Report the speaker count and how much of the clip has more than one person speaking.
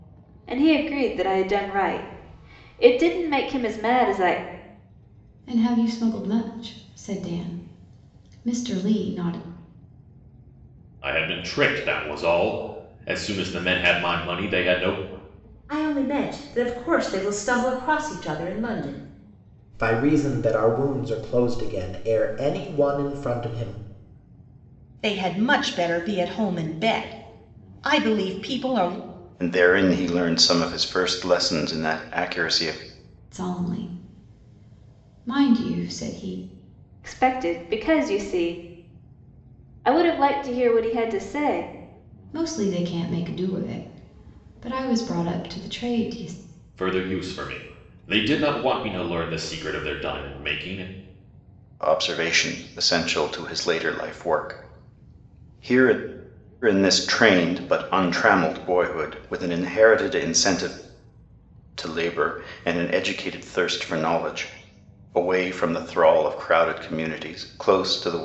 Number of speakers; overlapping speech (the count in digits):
7, no overlap